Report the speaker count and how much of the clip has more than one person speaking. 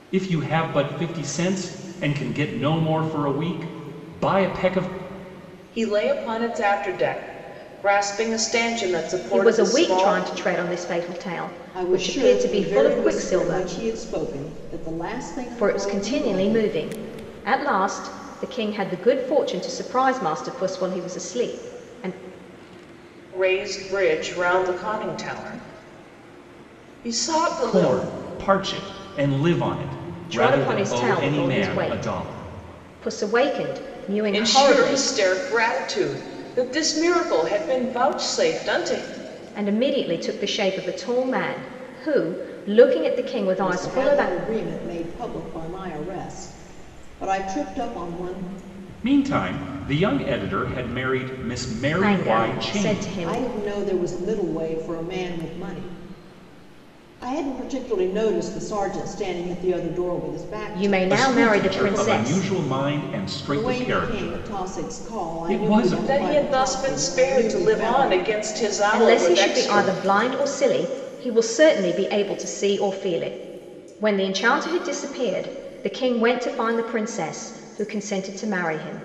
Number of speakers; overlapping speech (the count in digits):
4, about 22%